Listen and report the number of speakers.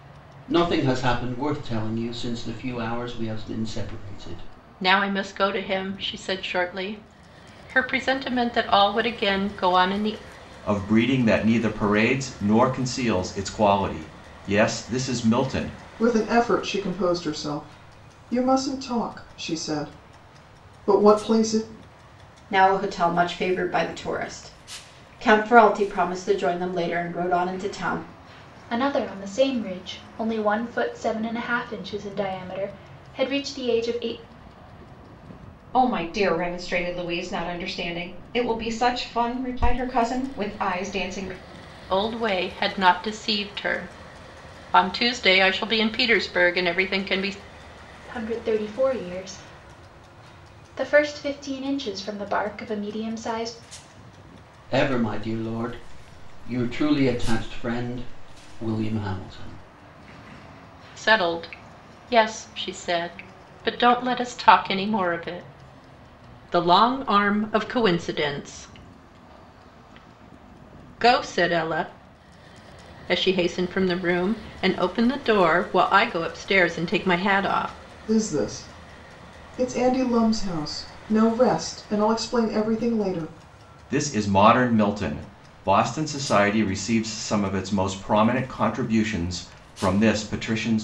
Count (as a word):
seven